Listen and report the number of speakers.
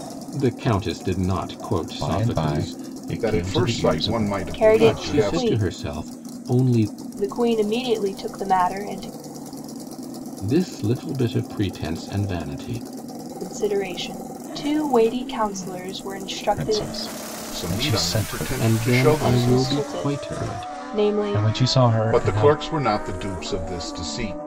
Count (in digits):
4